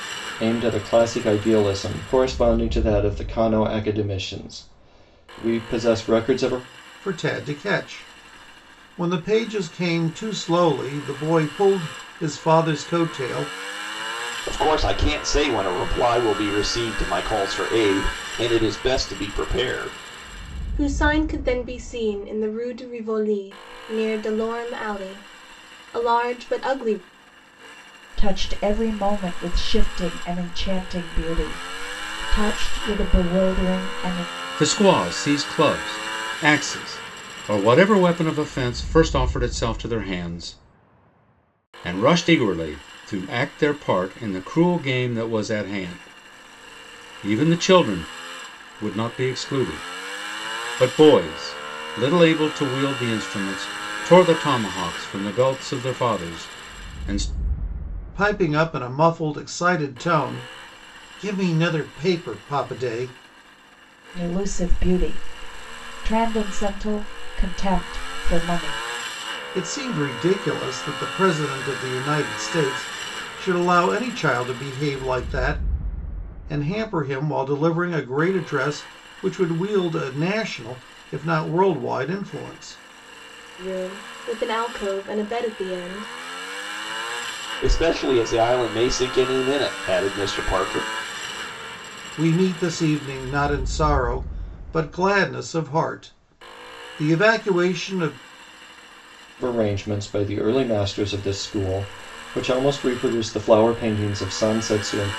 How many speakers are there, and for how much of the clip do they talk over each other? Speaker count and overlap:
6, no overlap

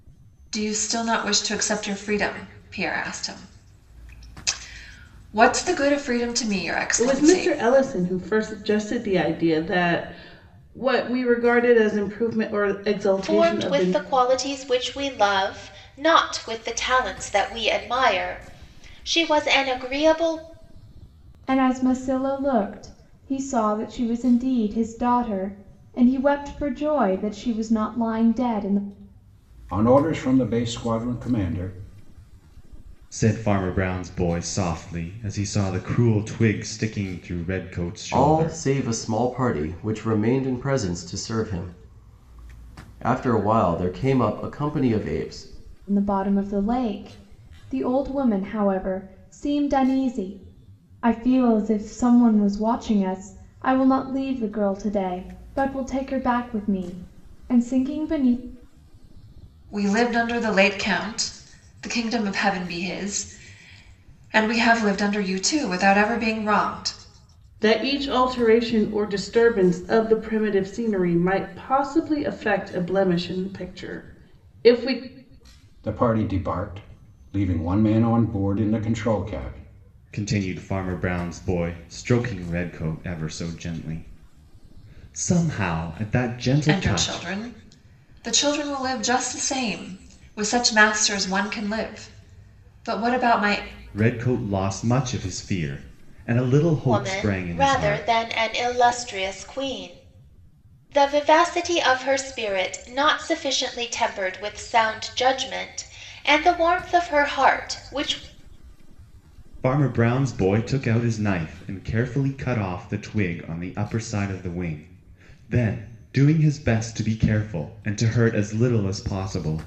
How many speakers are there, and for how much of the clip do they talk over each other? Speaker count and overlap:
7, about 3%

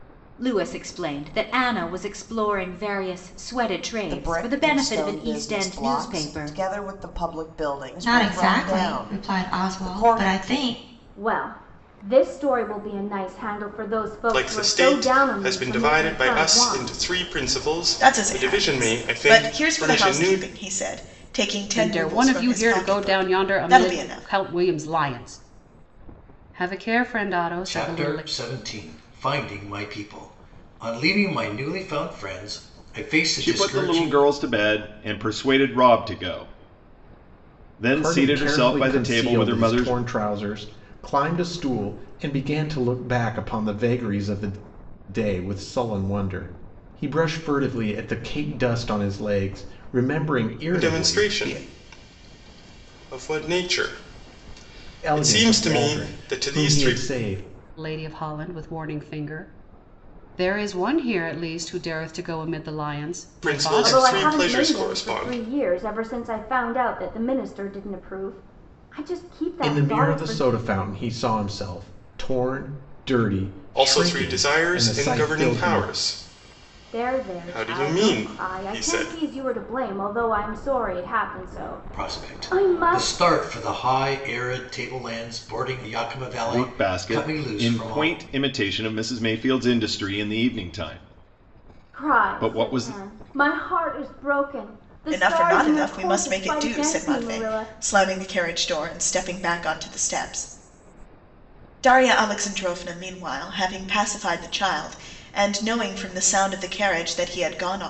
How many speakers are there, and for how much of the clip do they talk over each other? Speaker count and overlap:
10, about 31%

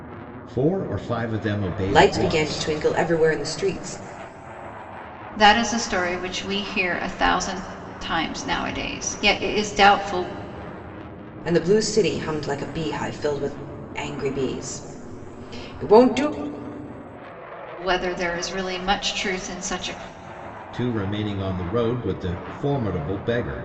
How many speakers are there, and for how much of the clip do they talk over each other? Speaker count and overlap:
3, about 3%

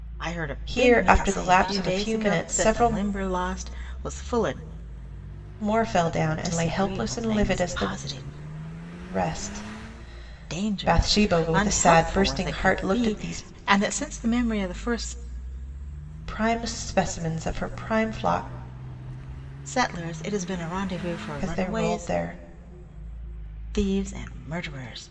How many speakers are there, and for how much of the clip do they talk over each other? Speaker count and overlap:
2, about 31%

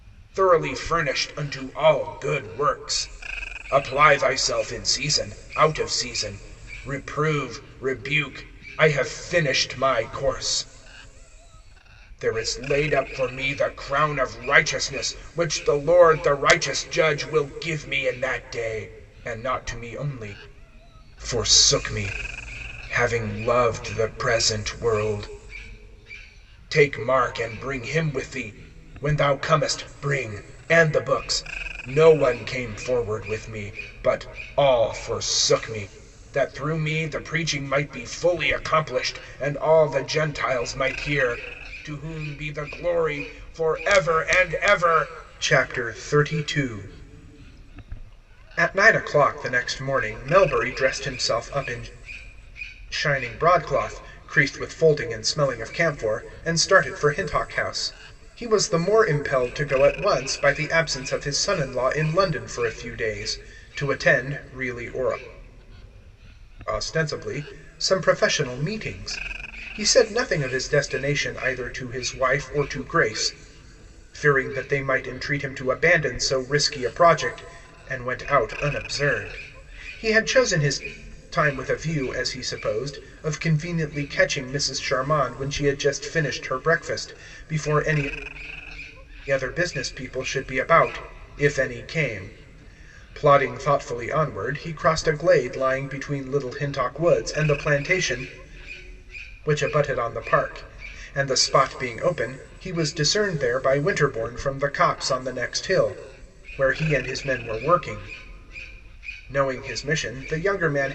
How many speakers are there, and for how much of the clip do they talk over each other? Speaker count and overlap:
1, no overlap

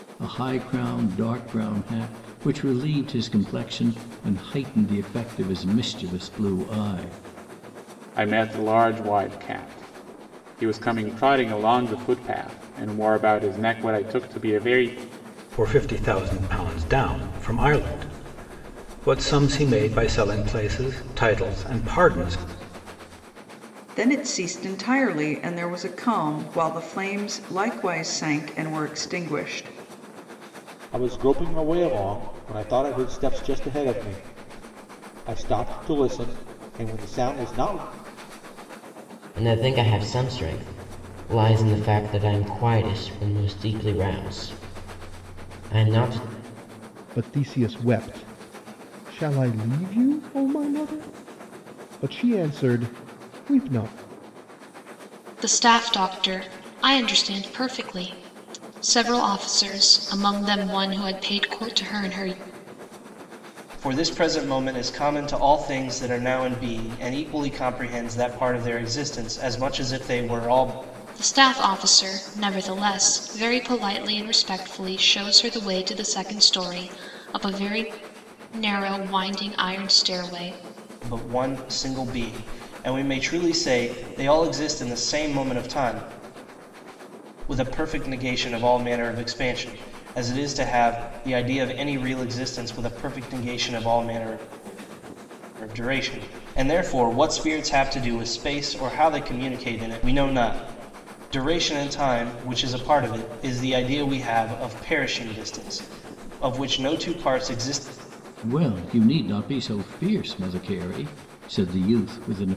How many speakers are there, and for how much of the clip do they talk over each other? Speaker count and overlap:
9, no overlap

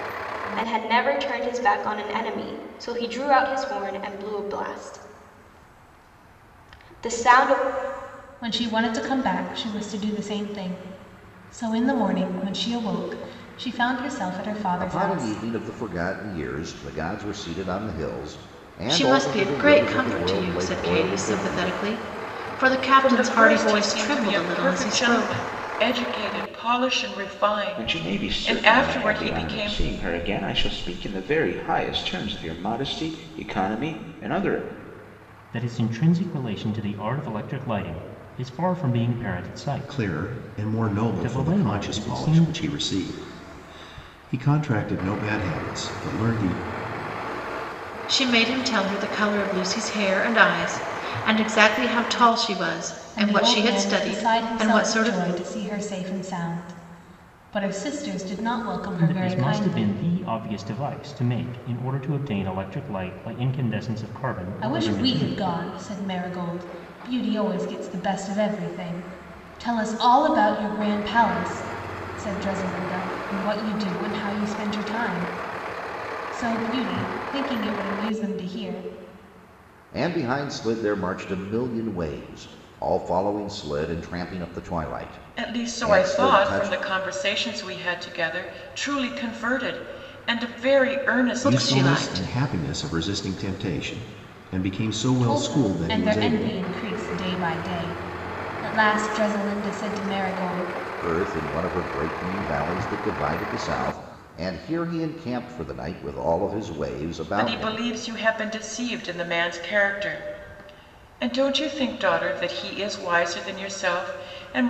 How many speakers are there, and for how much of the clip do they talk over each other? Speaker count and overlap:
8, about 17%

